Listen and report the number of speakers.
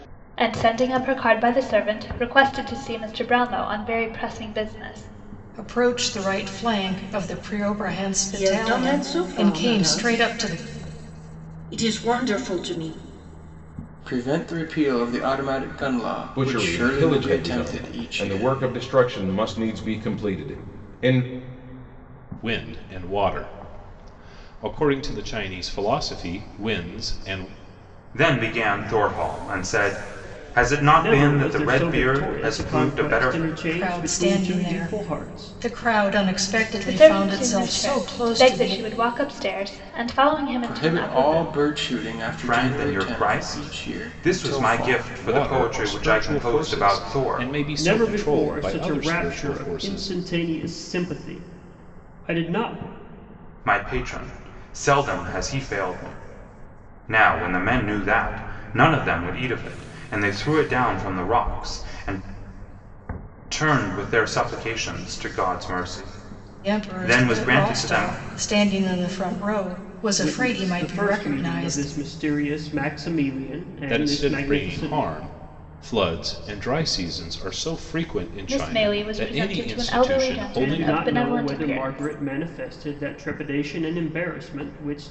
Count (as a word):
eight